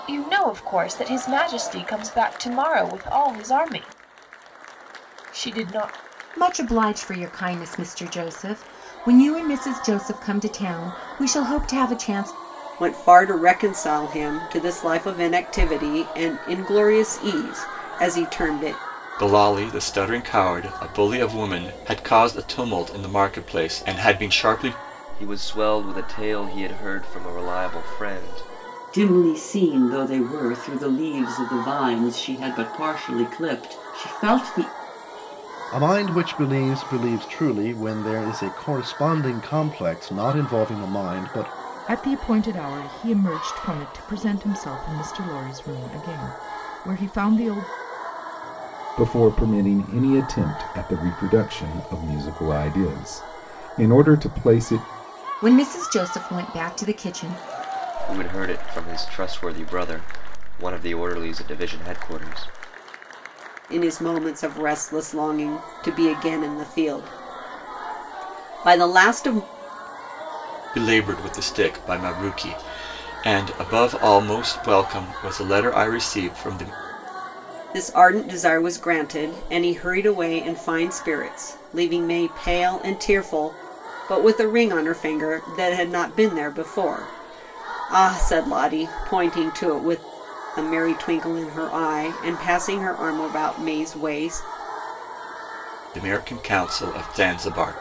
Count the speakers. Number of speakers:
9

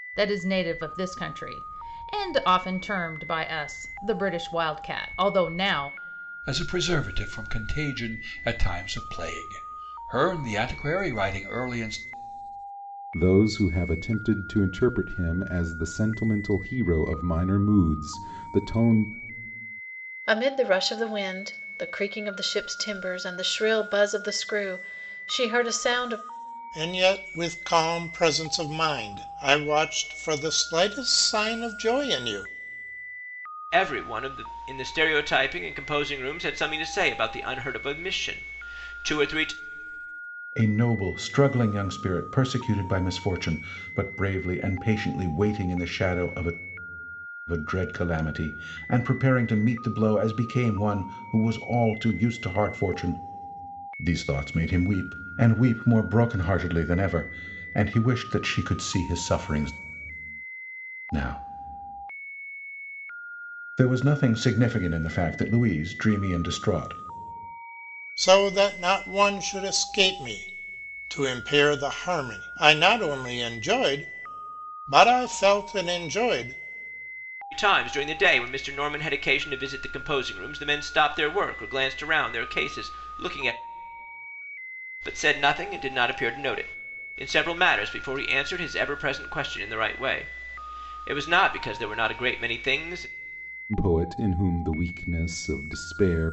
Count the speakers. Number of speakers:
7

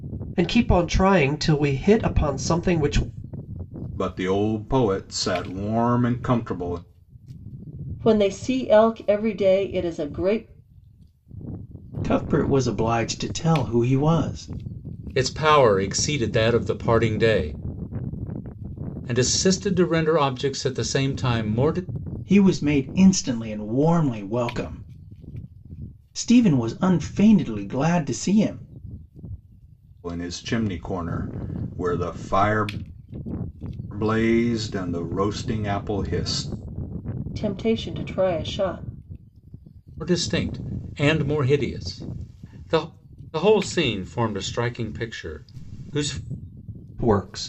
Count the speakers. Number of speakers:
5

